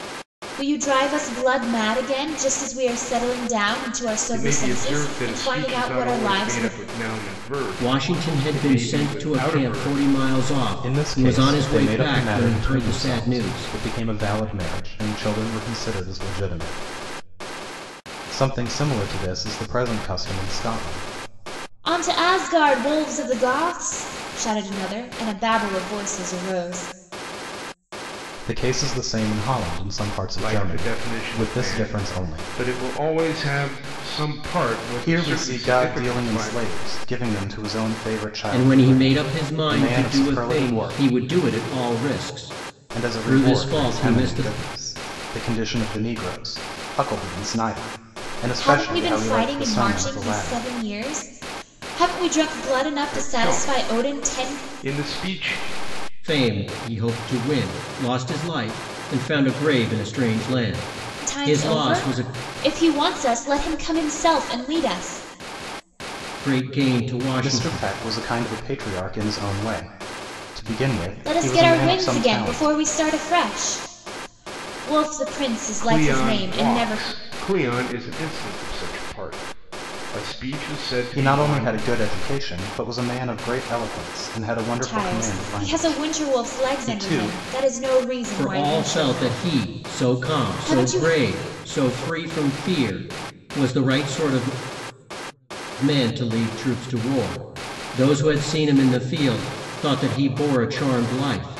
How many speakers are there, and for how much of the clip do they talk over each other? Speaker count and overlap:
four, about 30%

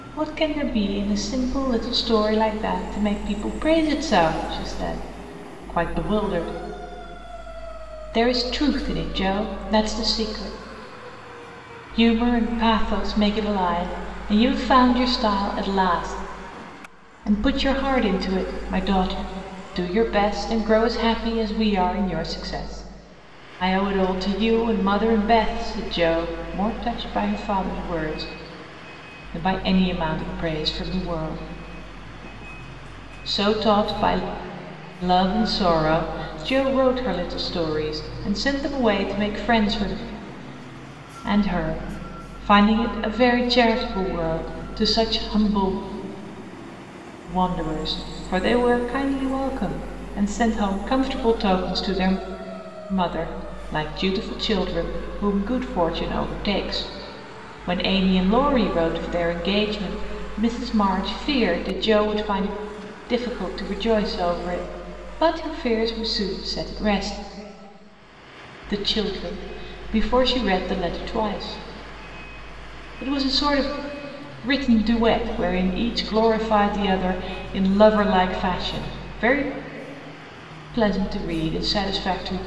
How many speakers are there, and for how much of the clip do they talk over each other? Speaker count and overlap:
one, no overlap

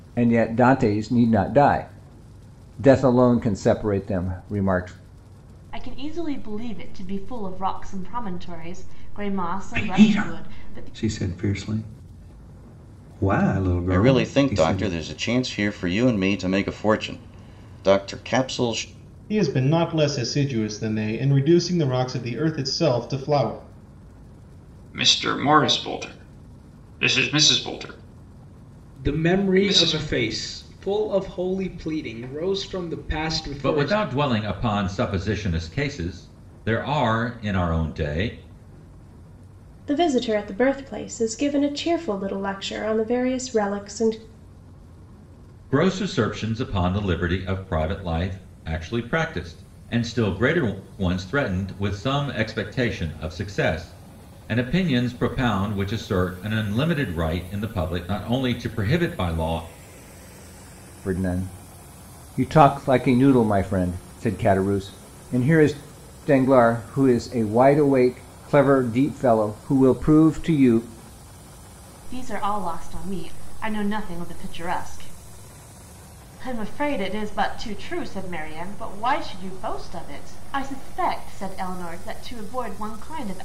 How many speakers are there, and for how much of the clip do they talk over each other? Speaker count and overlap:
nine, about 4%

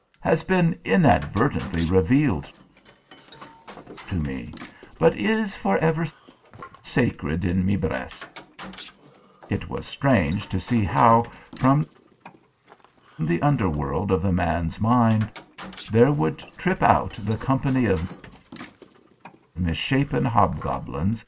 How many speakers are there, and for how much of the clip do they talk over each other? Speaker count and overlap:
one, no overlap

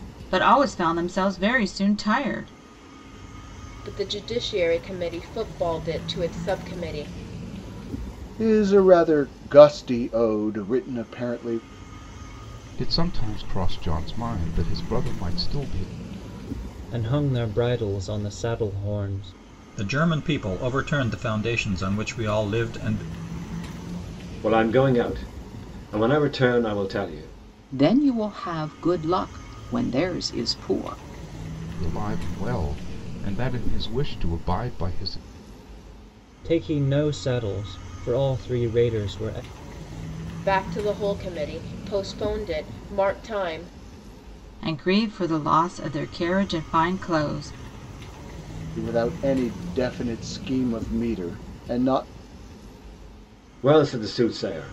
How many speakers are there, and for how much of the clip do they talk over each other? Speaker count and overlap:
eight, no overlap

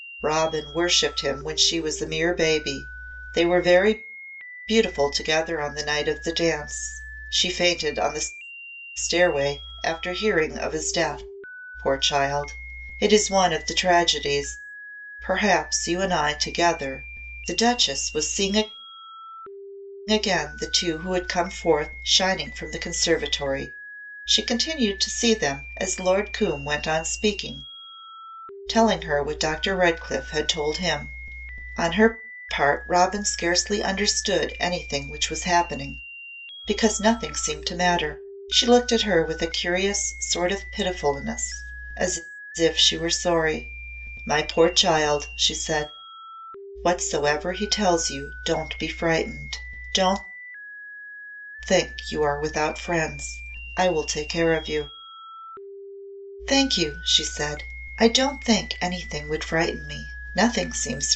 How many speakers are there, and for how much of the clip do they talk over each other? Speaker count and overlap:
one, no overlap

